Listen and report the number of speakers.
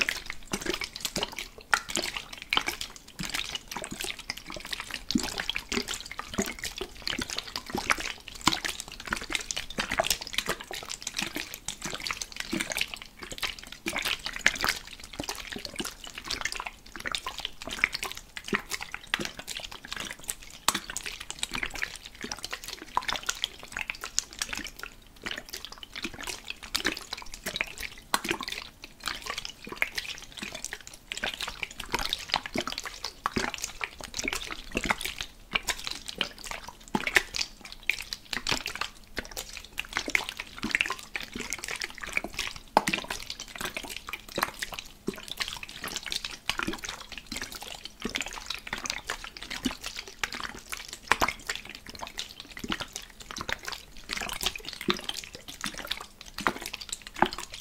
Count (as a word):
zero